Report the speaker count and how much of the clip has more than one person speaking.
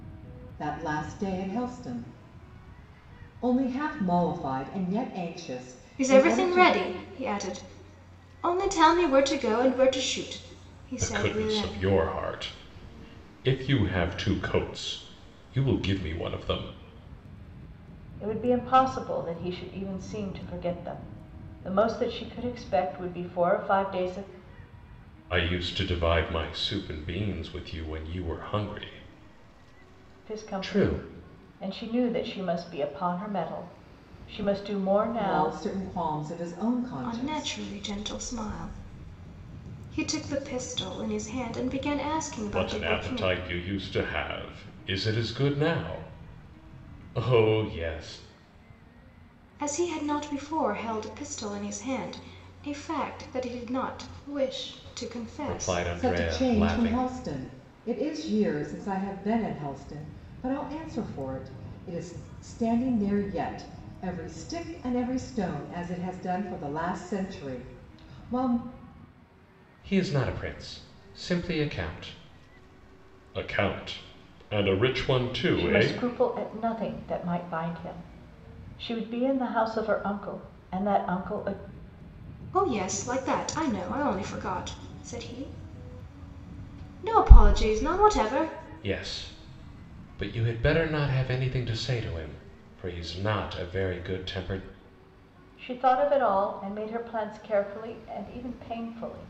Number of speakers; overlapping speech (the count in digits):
4, about 6%